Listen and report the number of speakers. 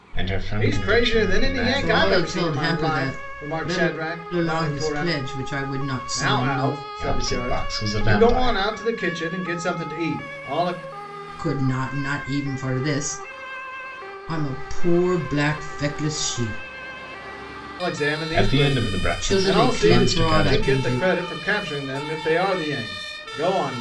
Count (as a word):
three